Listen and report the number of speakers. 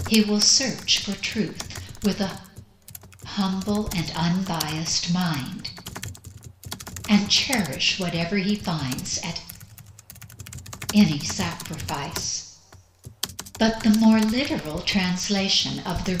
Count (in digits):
1